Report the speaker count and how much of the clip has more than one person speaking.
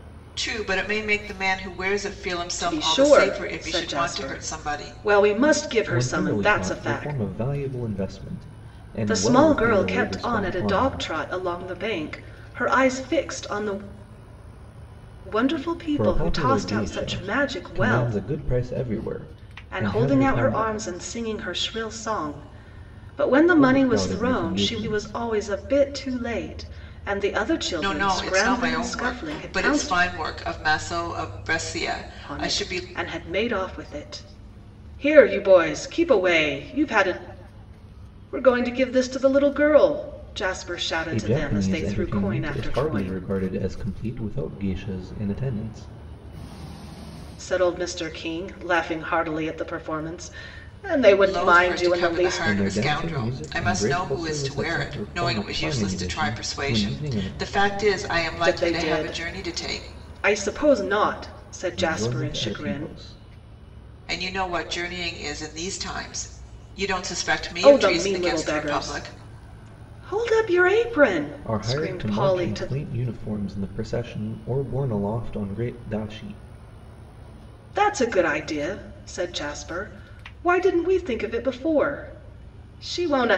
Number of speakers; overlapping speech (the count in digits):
3, about 33%